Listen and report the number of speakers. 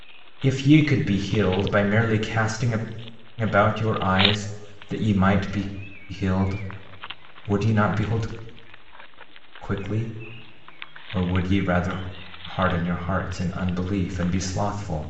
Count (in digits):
1